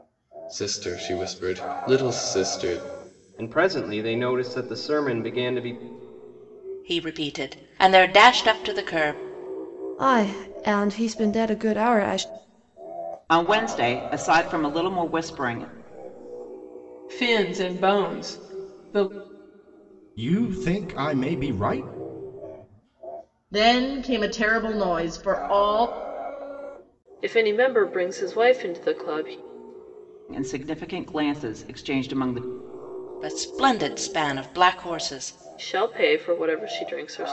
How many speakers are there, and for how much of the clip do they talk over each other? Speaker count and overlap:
9, no overlap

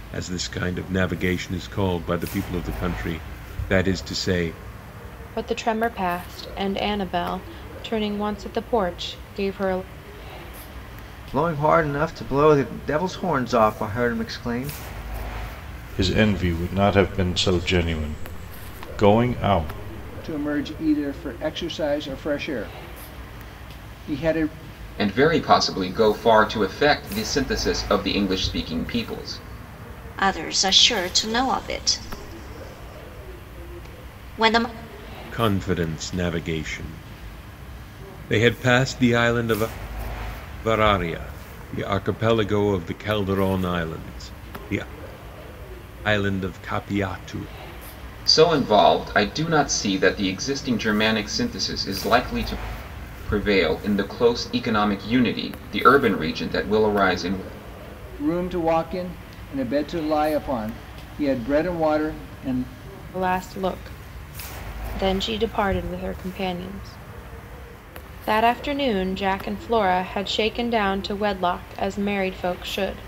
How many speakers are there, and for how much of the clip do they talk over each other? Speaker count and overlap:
7, no overlap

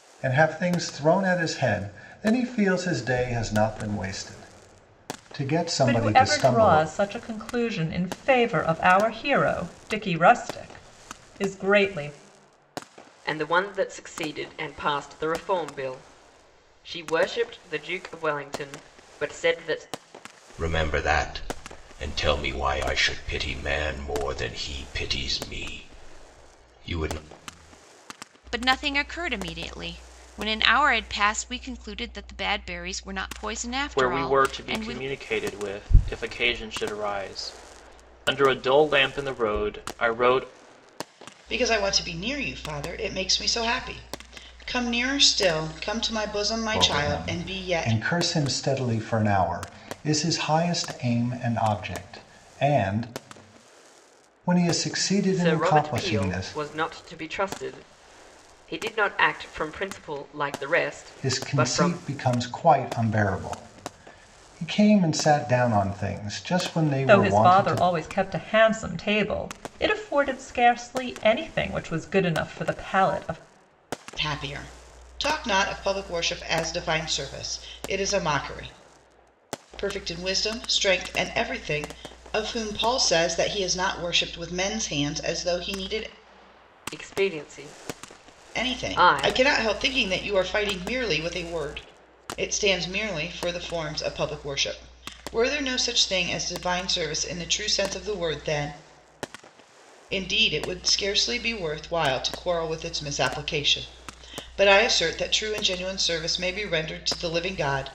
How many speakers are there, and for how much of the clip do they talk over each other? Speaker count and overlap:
7, about 7%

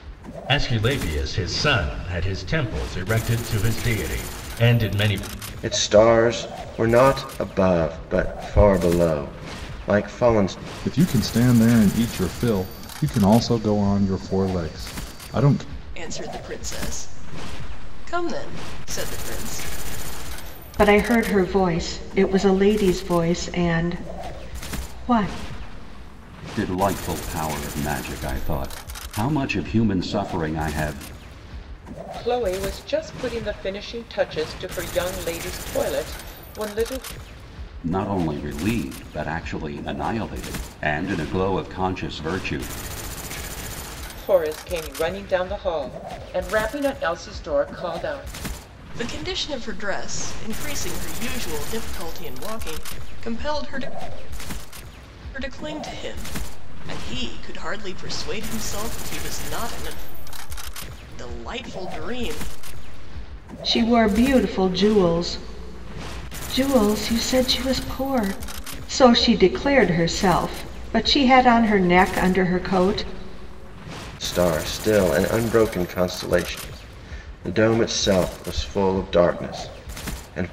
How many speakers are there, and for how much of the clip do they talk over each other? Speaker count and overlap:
7, no overlap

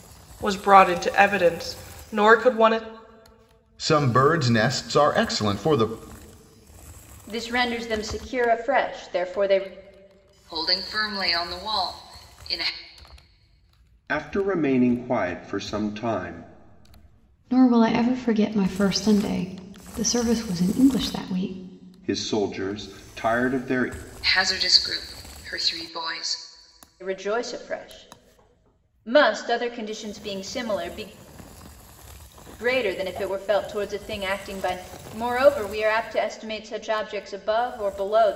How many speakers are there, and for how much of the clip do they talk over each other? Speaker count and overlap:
6, no overlap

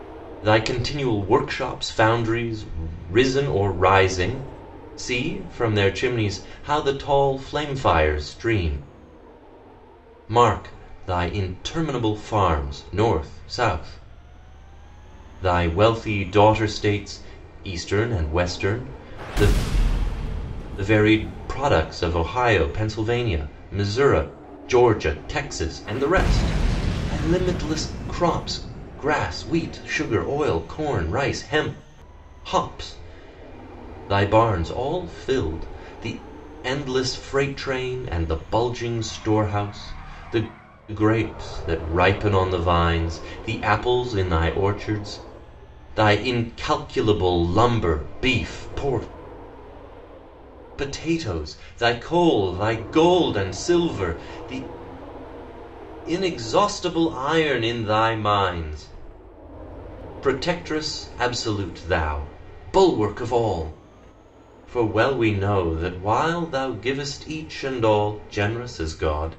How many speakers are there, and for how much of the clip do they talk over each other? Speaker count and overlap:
1, no overlap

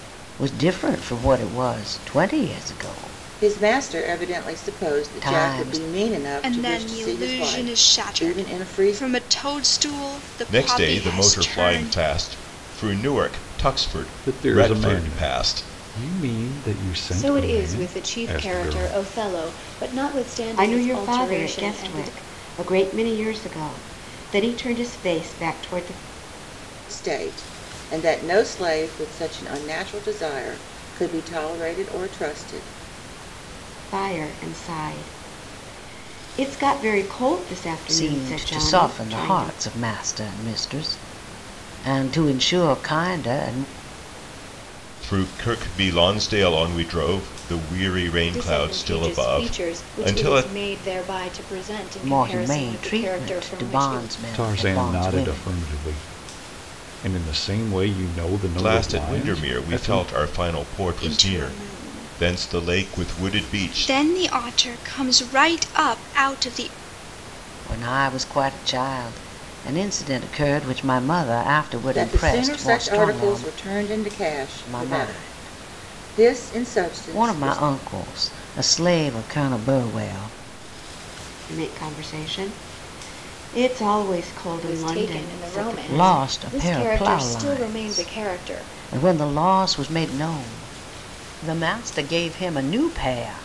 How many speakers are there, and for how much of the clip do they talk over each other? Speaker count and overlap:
7, about 34%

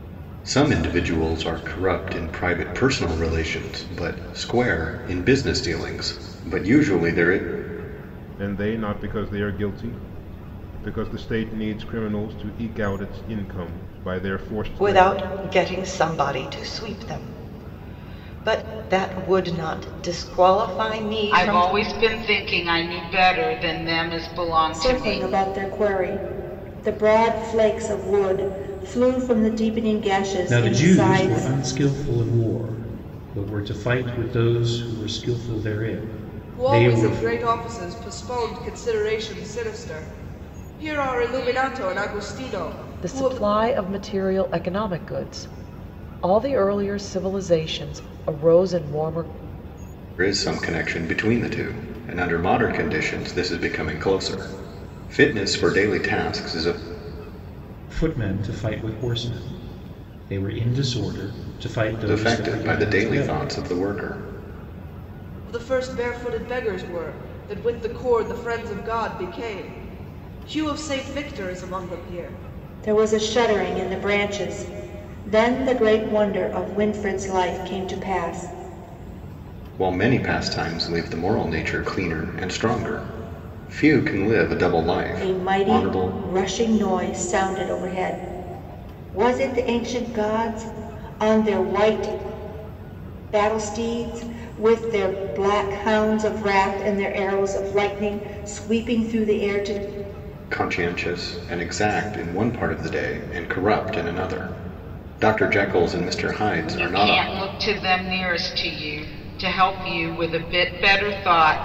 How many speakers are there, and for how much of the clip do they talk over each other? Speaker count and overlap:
8, about 6%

